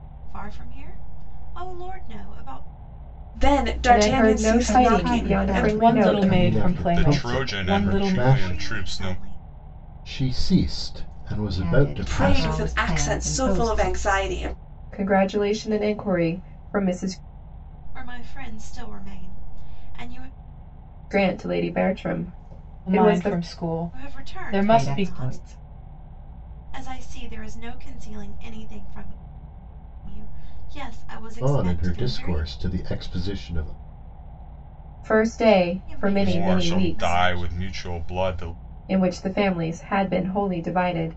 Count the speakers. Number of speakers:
7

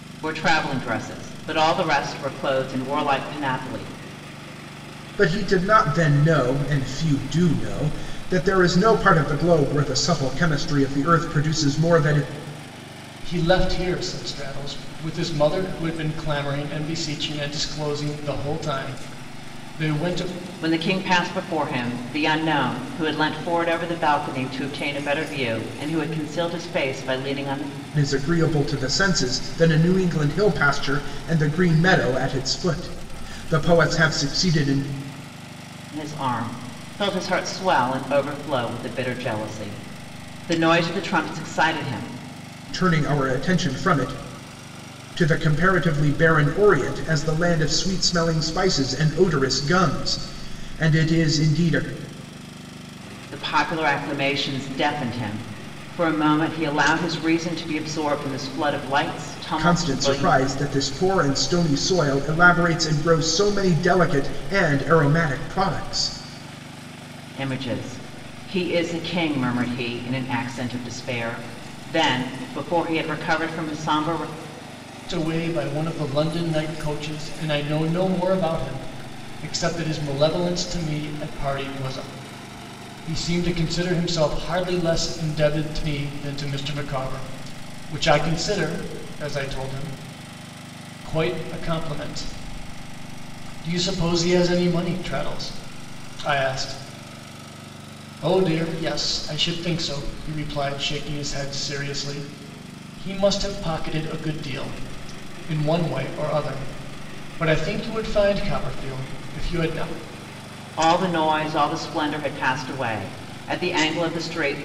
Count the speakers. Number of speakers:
3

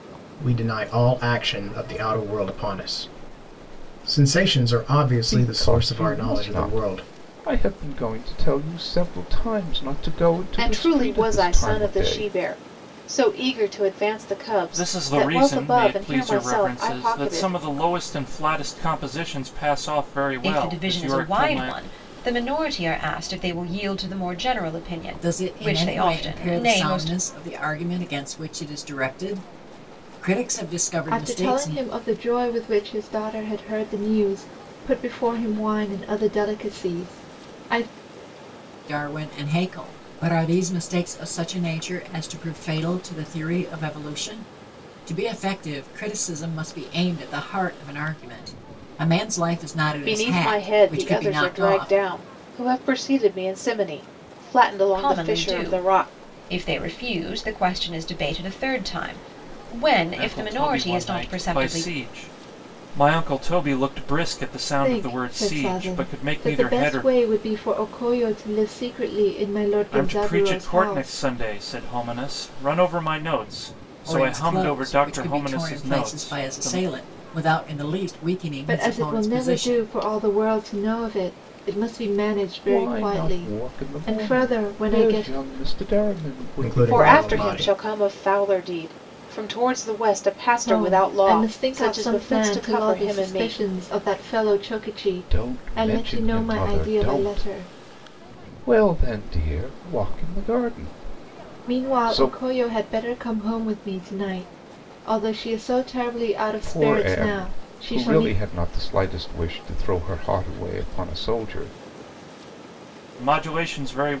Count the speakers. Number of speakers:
7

